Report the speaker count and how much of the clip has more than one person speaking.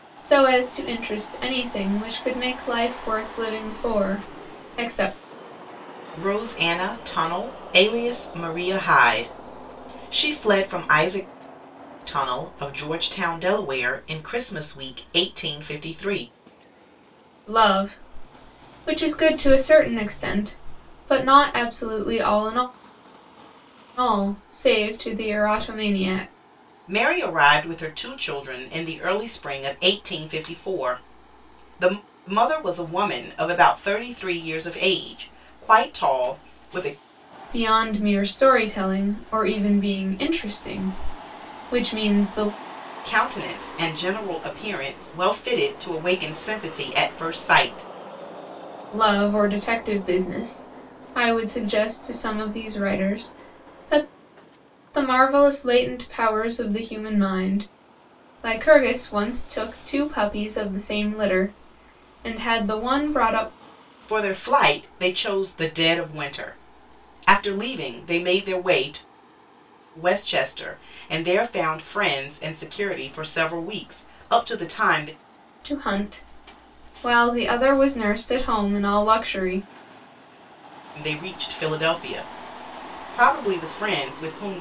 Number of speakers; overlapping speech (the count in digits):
2, no overlap